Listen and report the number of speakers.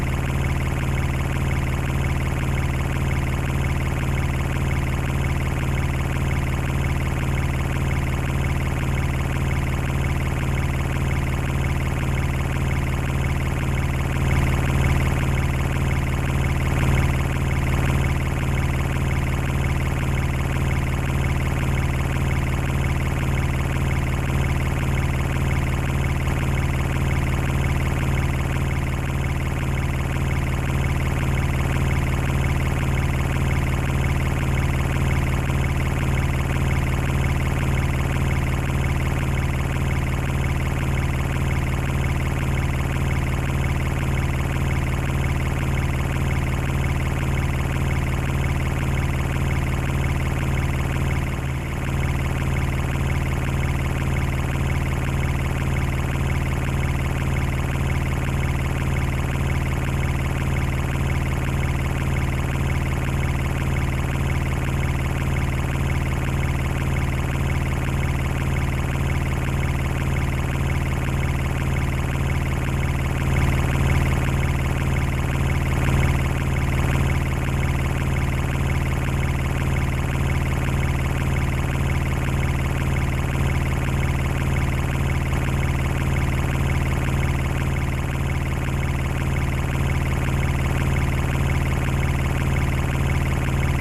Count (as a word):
zero